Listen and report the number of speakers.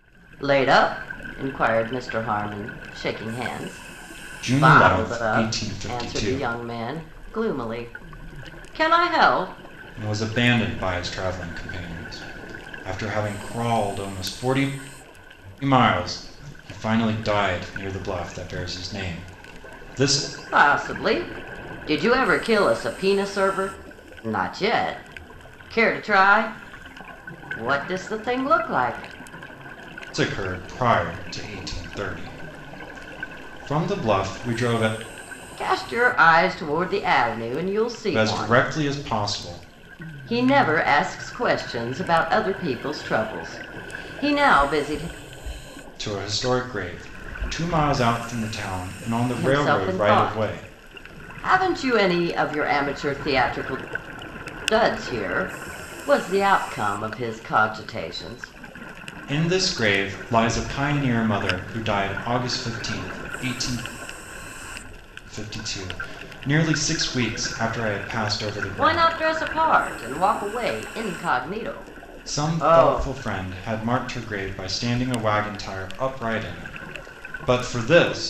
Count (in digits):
2